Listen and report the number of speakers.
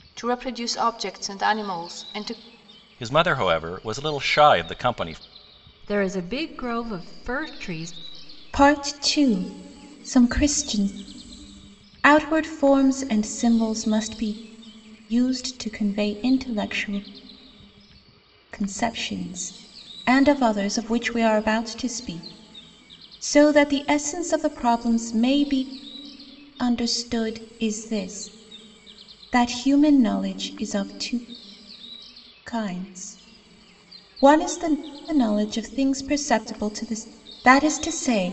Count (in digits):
4